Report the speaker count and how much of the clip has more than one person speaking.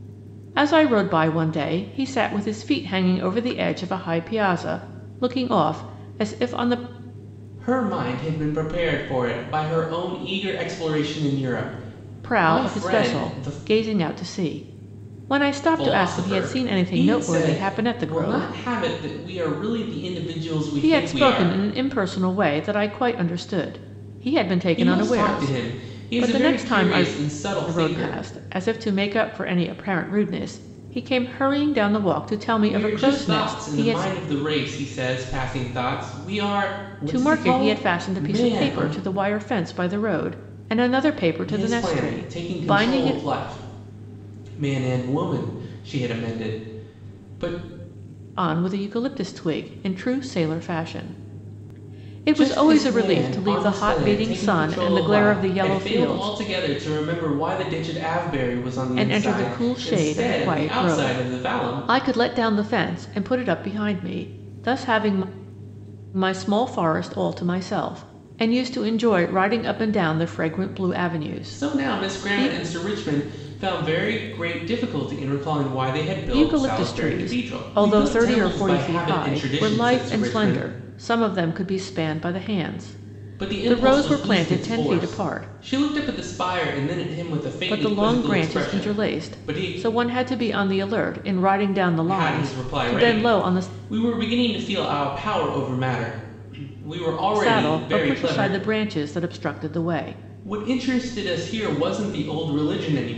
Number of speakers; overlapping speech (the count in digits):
2, about 32%